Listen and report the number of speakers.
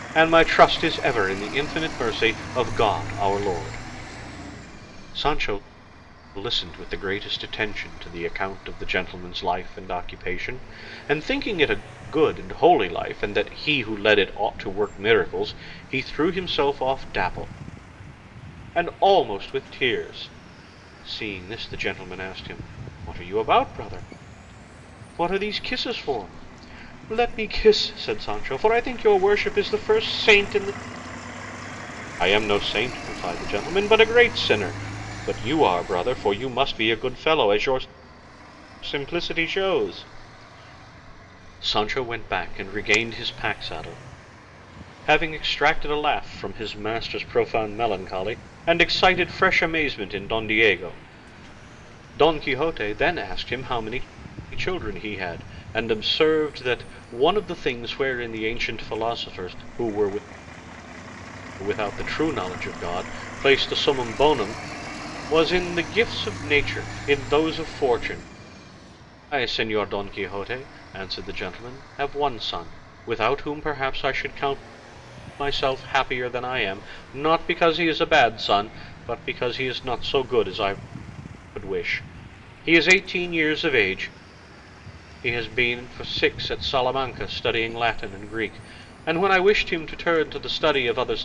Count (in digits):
1